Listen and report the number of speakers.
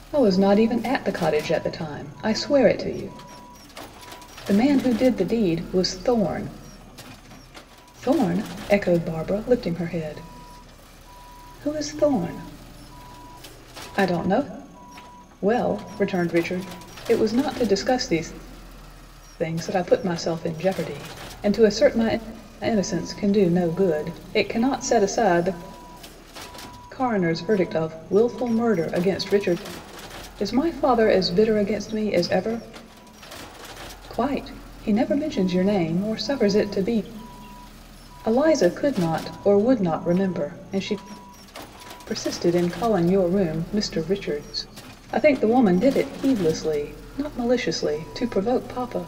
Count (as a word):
one